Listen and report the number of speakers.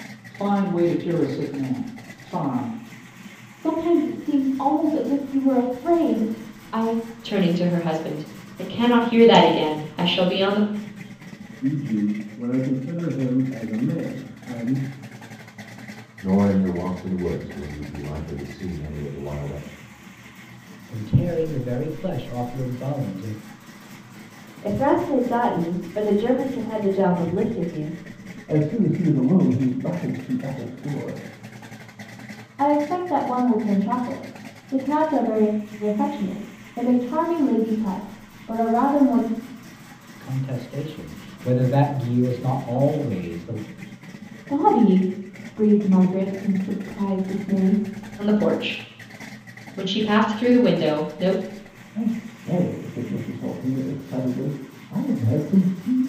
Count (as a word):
nine